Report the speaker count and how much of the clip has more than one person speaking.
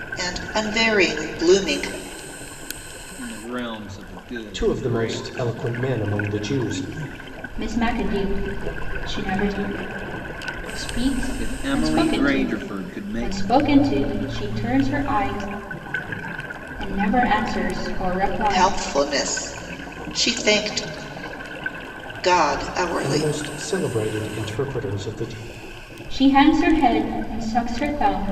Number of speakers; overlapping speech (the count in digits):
4, about 11%